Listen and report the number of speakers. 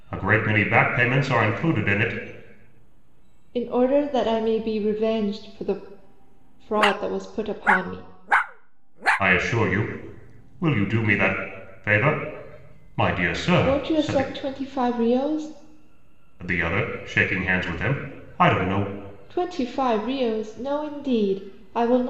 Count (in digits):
2